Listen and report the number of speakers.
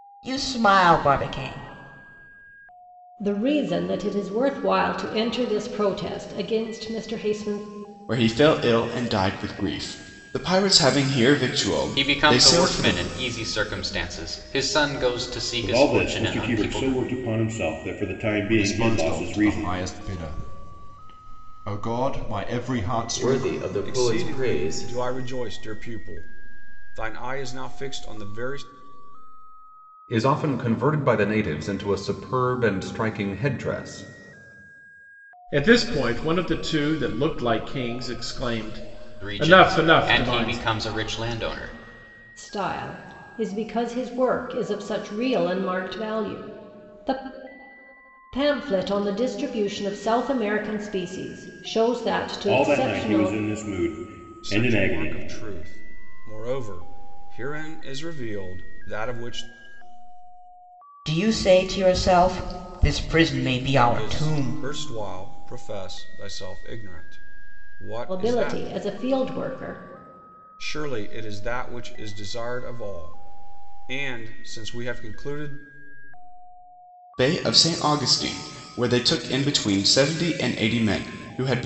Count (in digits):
10